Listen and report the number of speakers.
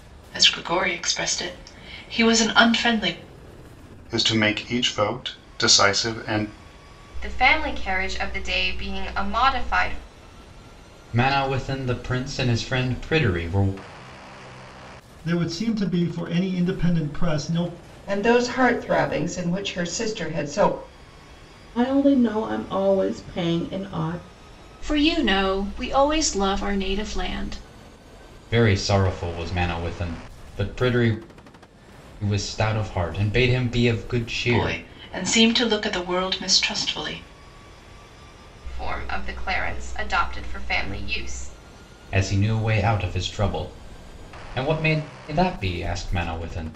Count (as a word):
eight